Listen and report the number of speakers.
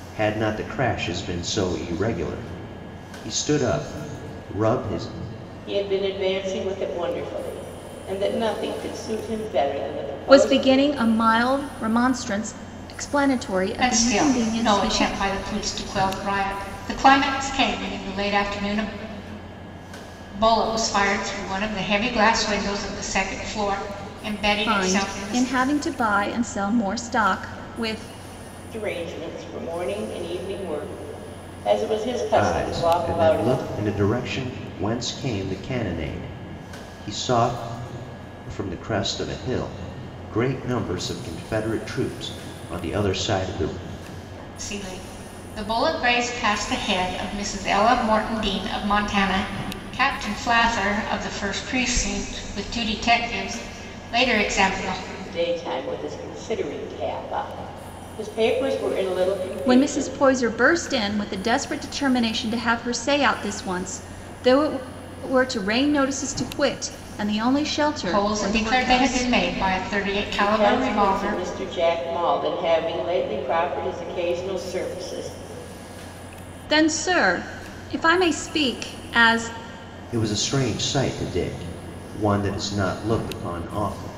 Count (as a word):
four